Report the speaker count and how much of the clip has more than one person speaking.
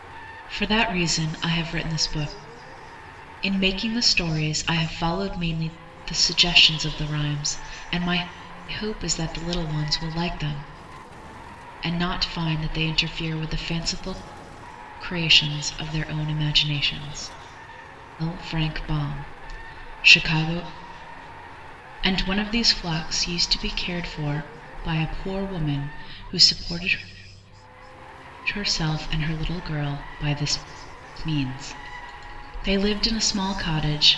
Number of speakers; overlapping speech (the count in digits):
1, no overlap